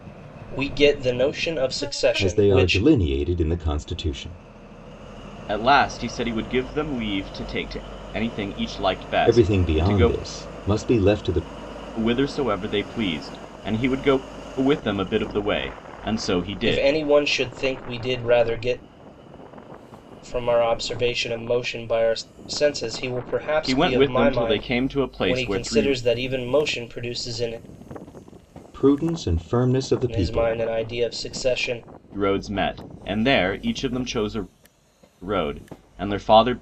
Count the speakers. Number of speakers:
3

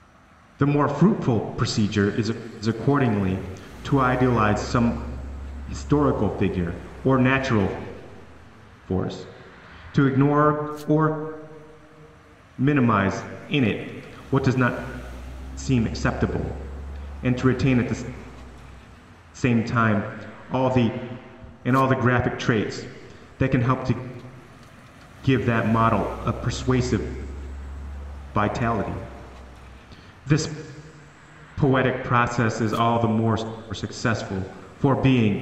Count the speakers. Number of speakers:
1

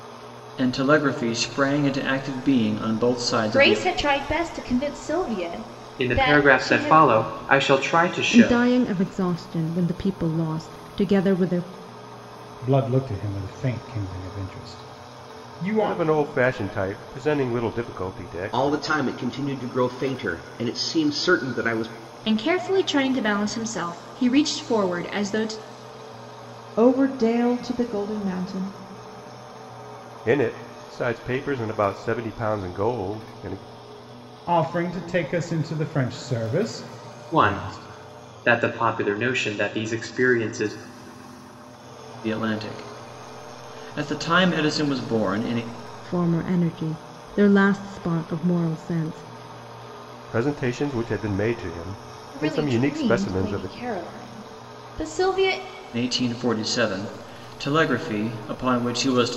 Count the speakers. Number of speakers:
9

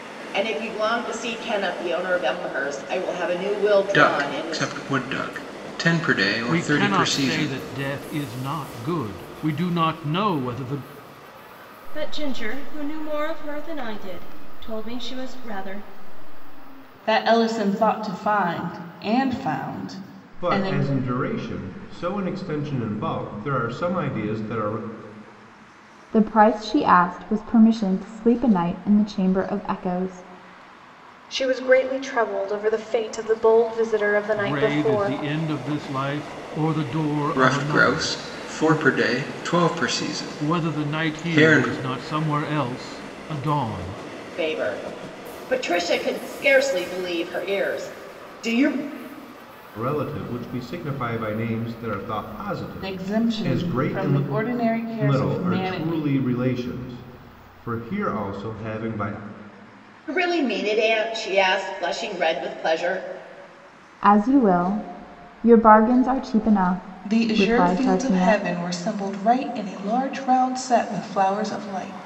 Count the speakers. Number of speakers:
8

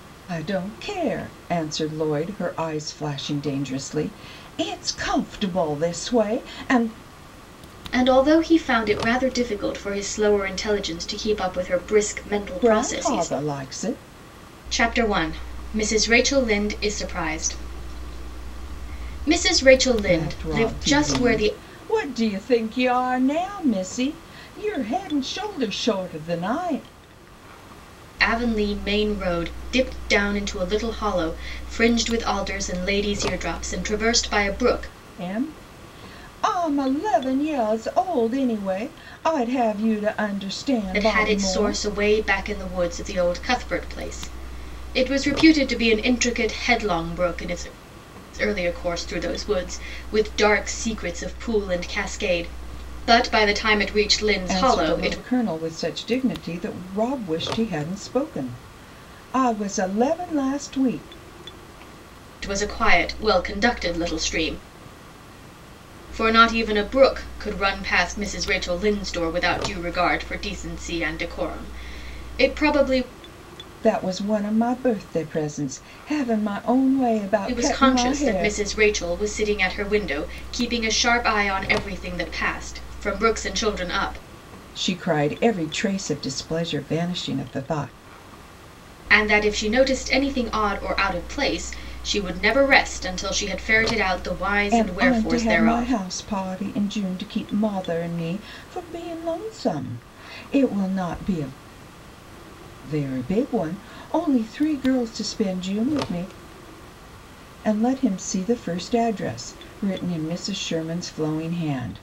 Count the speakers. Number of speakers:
2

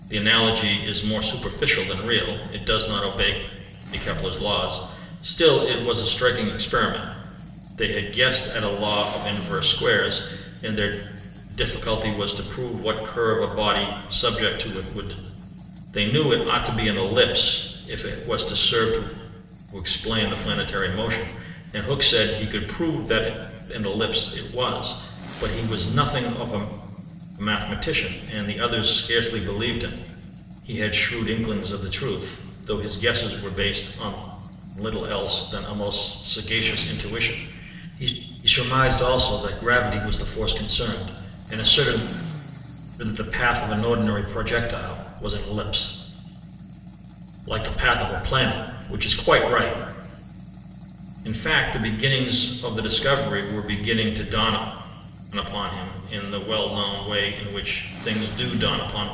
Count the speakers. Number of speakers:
1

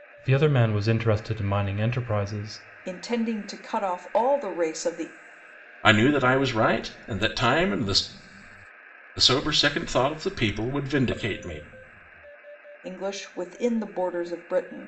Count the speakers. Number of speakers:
3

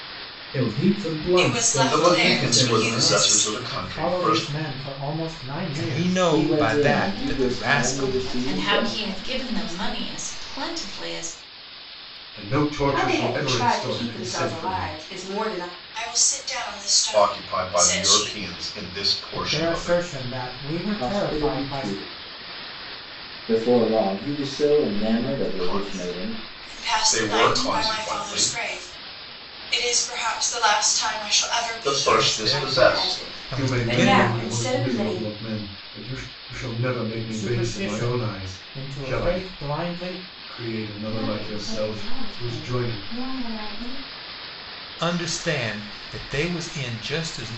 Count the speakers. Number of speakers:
10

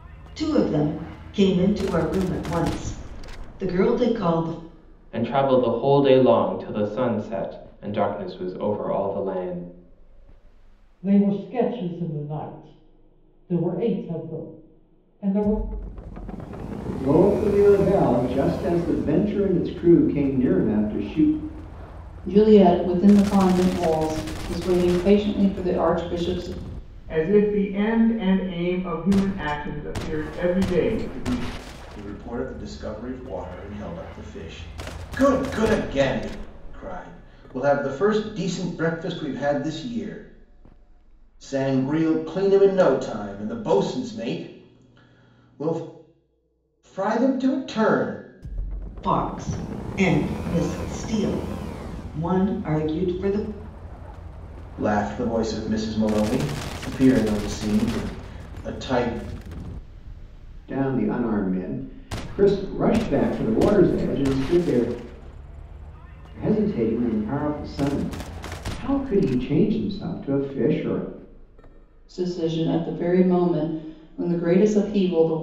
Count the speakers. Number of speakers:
7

